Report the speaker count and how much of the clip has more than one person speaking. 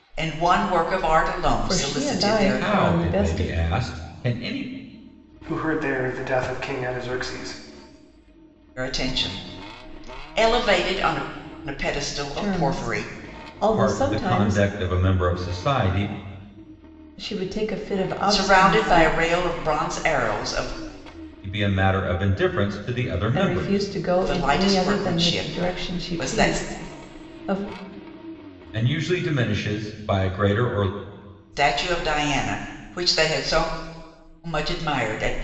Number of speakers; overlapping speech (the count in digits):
4, about 21%